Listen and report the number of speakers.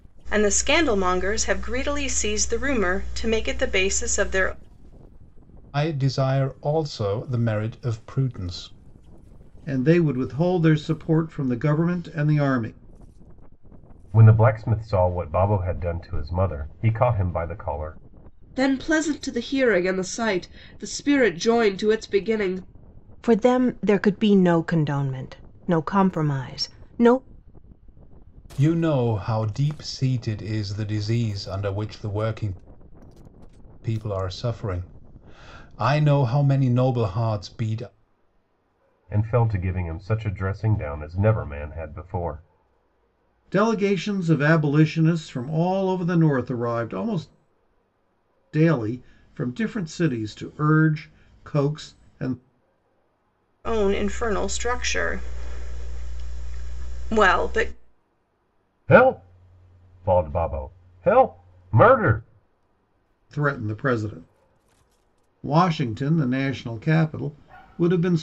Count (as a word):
six